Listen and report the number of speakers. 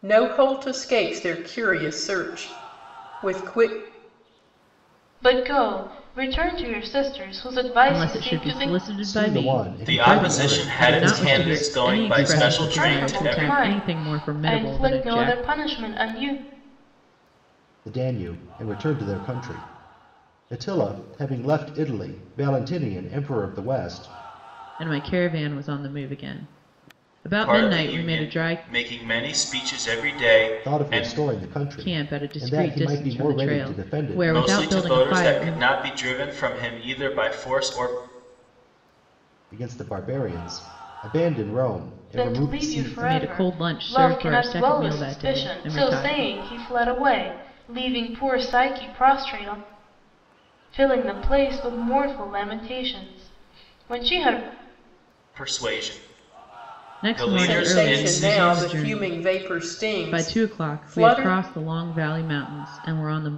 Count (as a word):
five